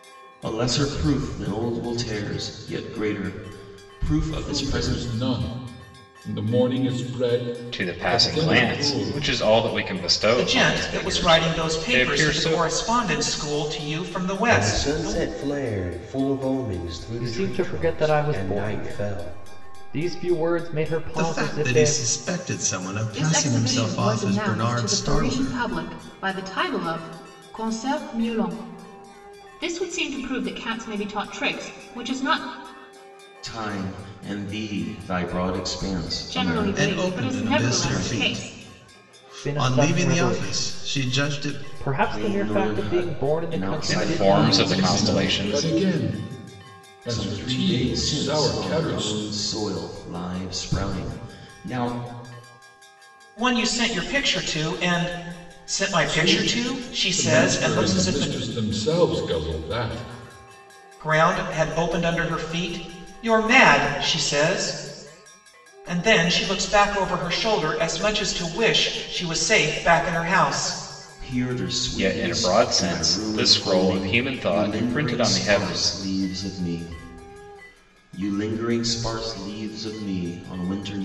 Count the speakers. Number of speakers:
eight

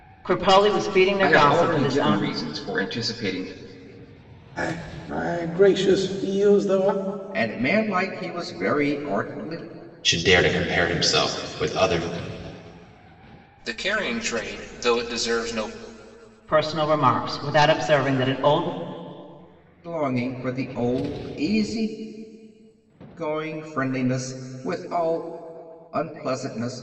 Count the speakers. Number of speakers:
six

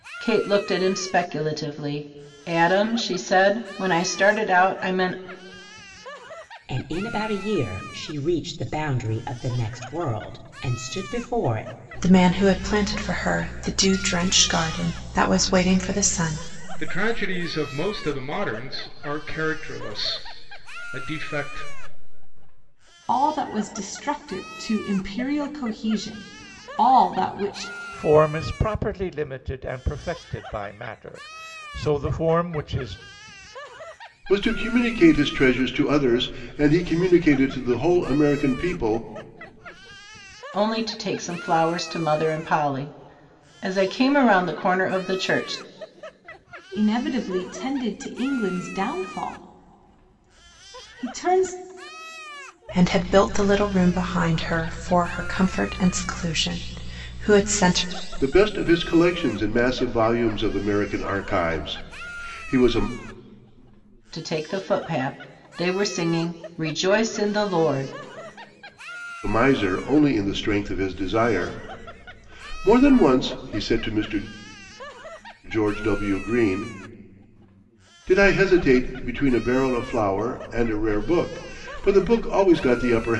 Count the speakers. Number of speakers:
seven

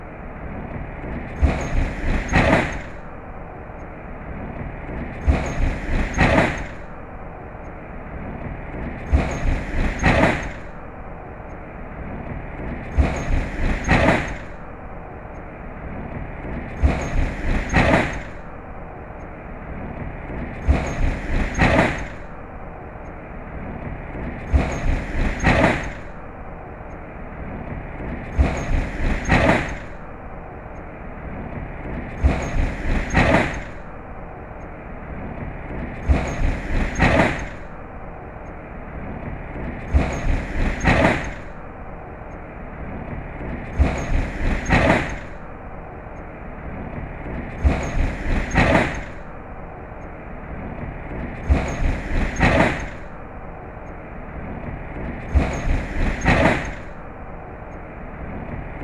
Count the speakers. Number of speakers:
zero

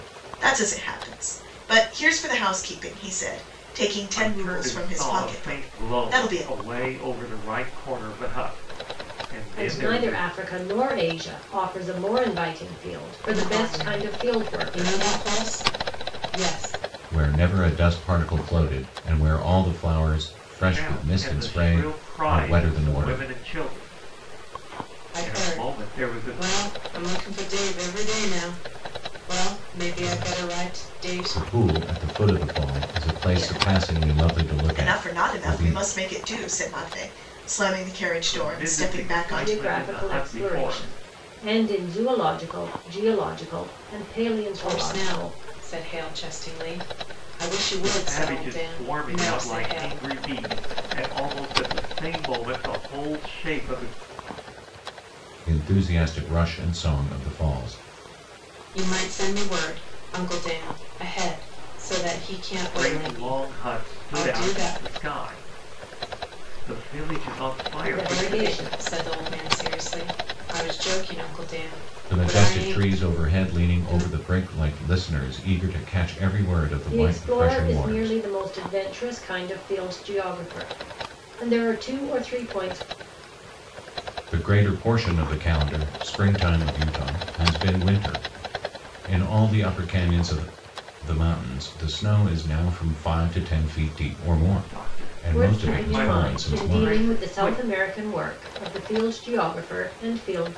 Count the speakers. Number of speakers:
five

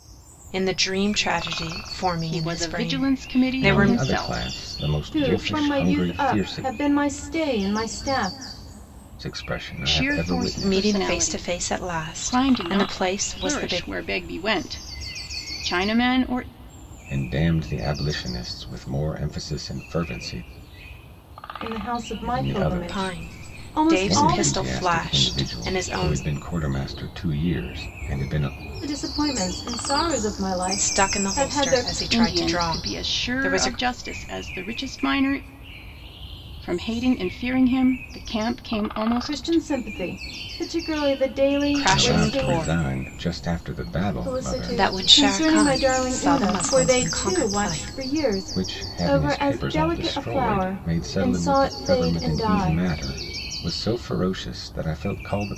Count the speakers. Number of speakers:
four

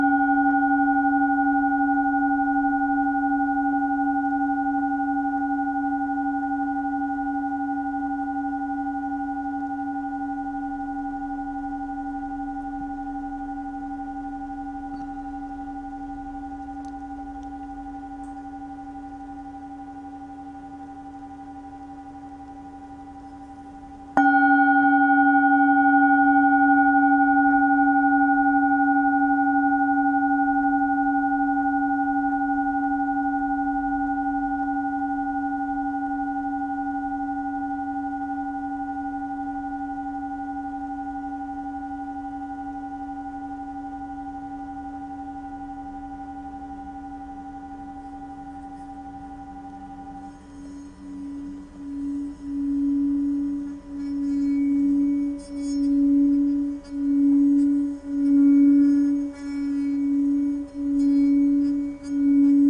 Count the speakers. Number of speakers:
zero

